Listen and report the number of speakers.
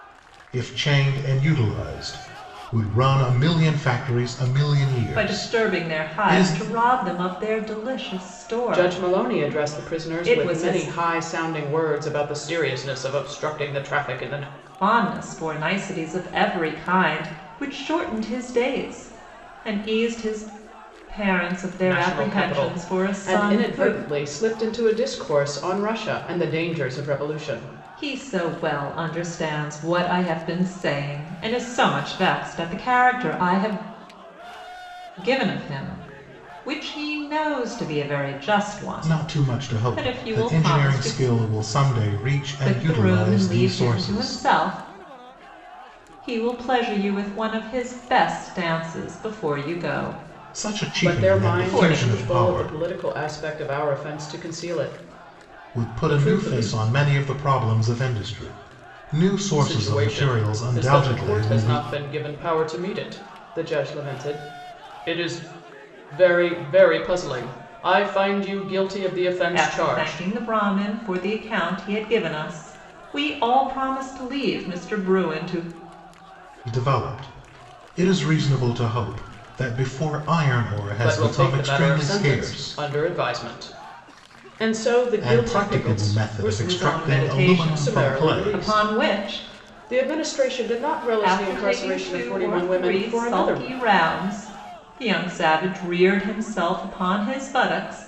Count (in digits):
3